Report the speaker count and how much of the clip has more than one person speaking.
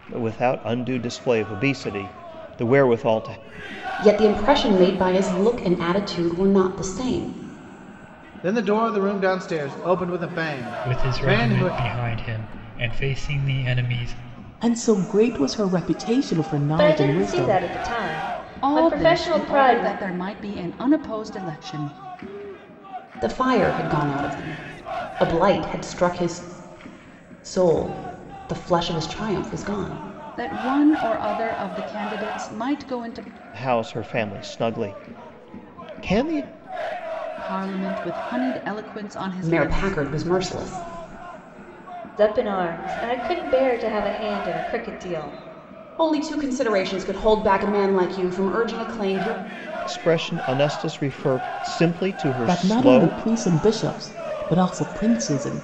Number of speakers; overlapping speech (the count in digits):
7, about 8%